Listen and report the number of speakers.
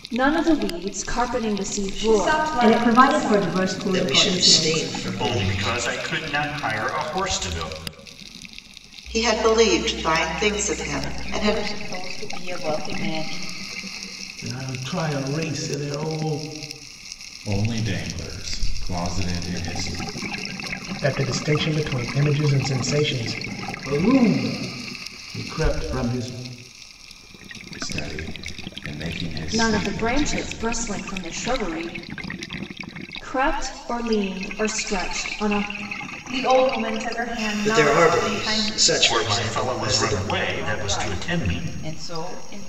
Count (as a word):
ten